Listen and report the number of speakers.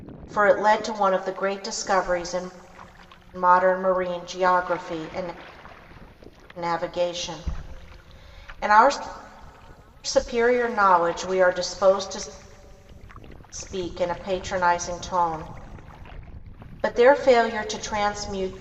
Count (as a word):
one